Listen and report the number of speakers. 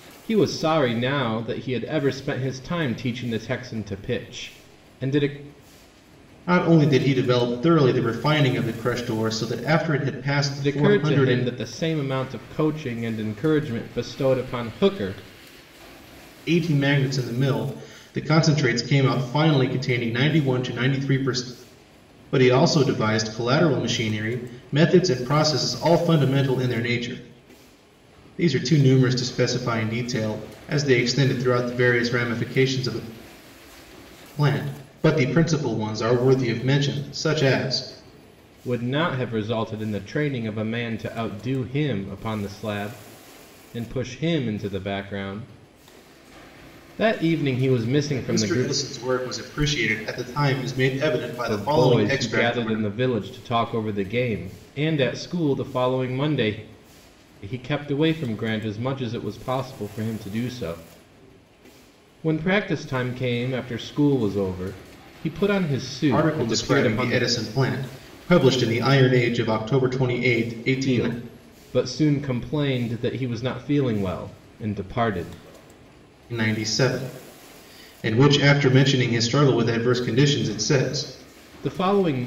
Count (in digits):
2